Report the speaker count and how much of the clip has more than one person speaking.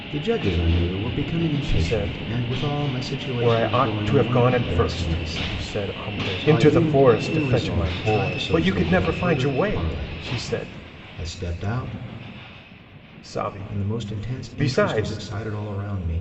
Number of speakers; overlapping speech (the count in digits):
2, about 63%